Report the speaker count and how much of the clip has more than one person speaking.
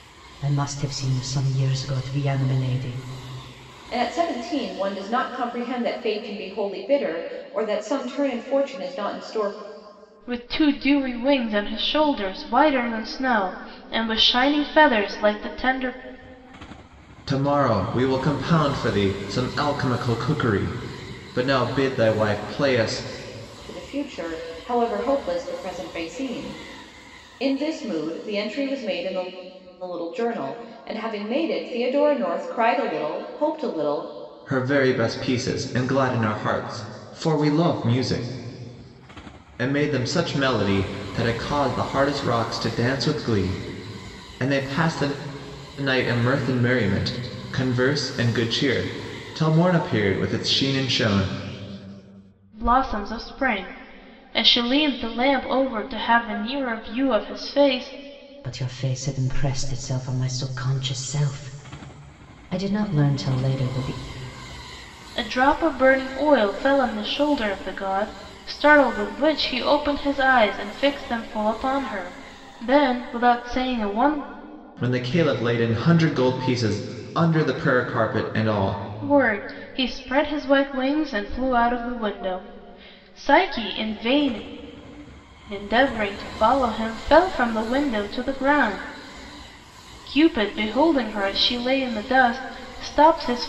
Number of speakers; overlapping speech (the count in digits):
4, no overlap